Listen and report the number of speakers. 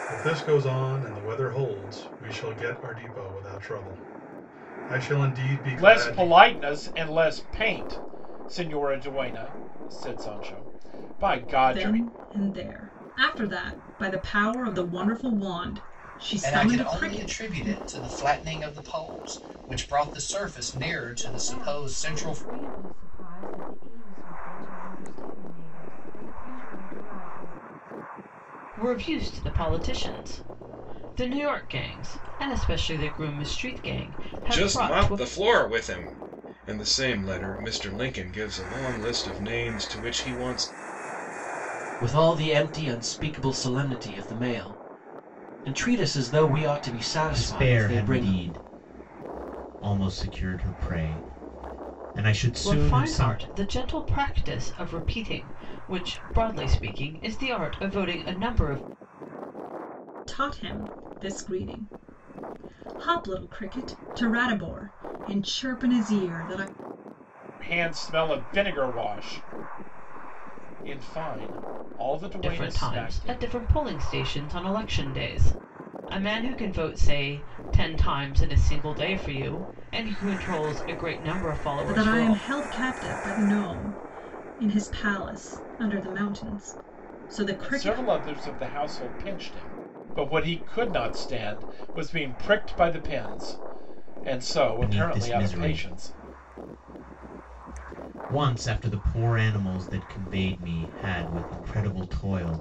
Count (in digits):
9